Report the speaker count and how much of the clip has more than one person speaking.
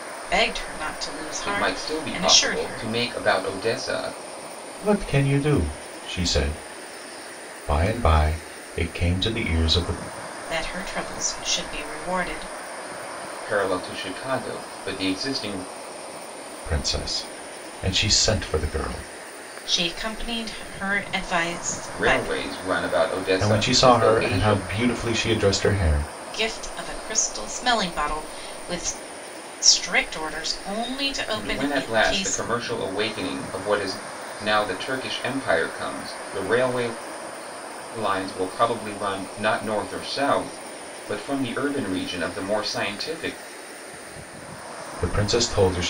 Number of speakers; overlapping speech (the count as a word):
three, about 10%